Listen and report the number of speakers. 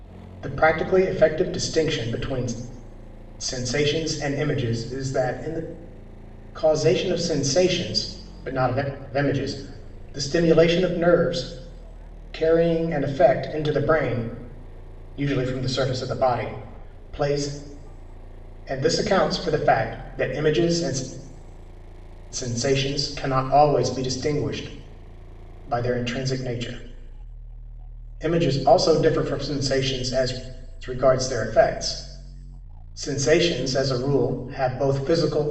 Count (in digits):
1